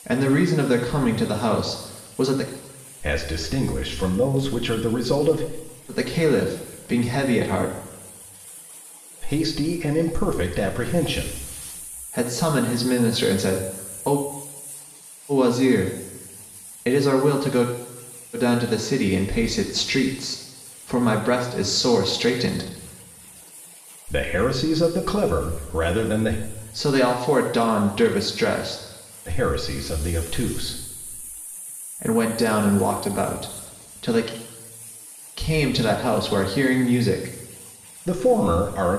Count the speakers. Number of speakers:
2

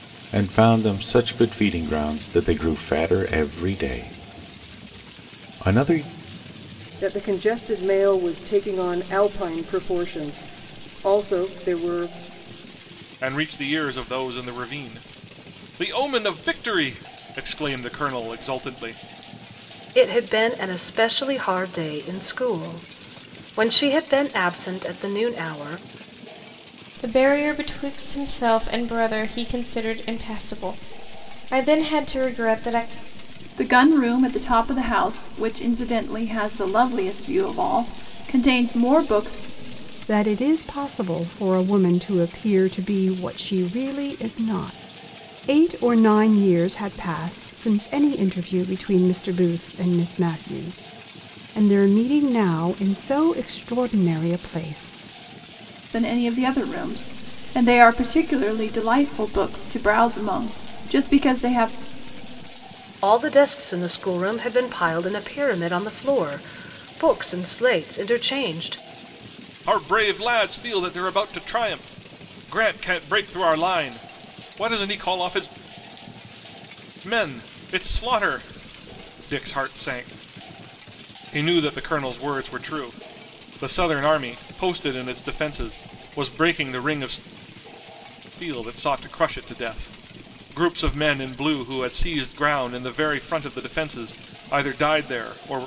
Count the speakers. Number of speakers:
7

